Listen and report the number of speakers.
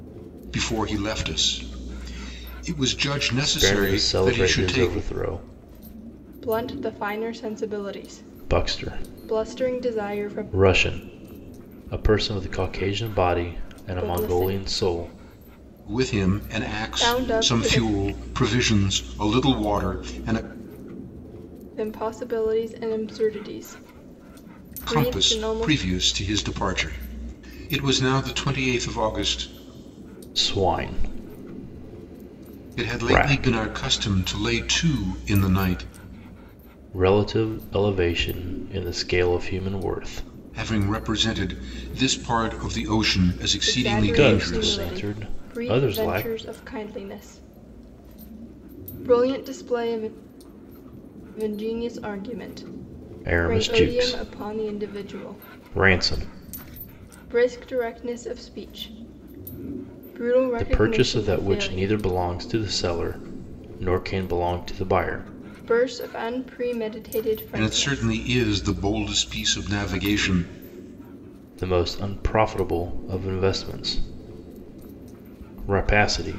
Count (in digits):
3